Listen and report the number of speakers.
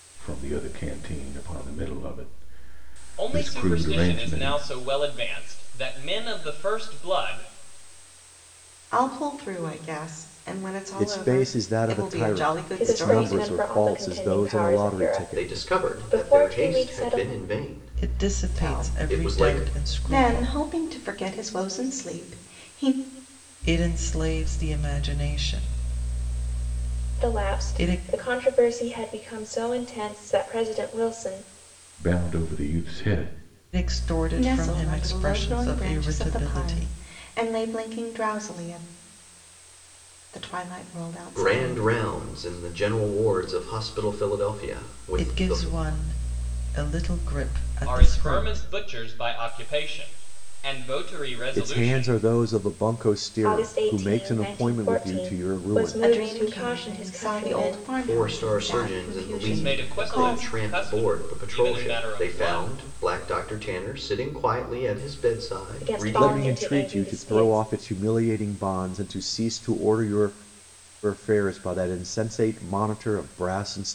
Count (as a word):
seven